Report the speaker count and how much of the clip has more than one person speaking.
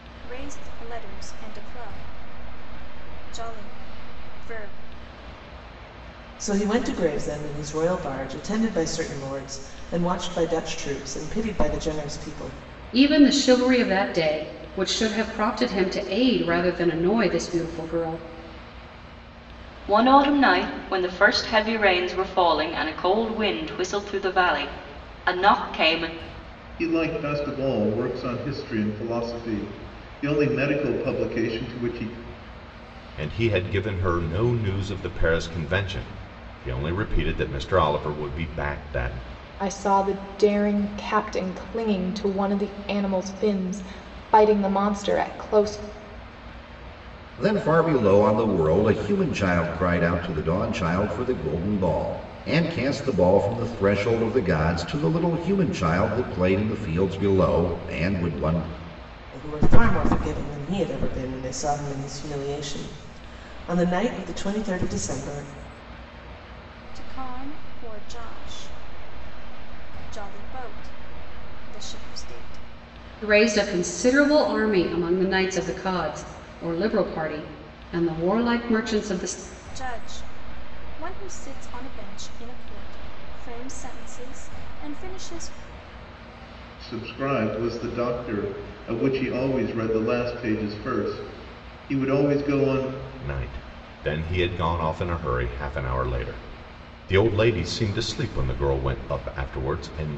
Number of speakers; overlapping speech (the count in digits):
8, no overlap